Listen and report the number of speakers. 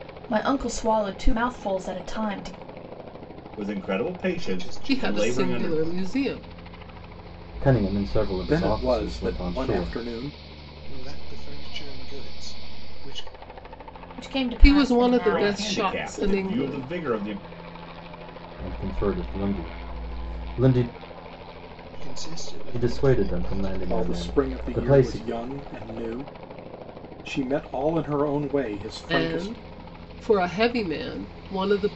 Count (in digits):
6